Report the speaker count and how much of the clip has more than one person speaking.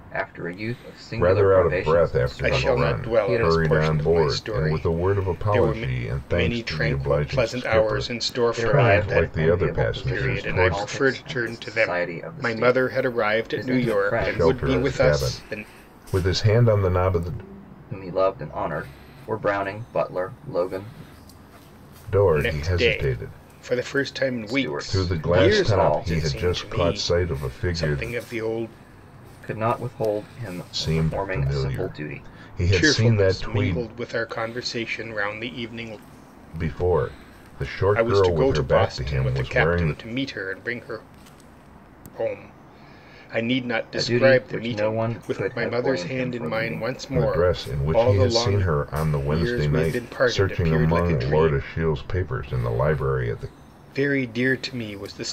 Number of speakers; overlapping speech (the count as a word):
three, about 54%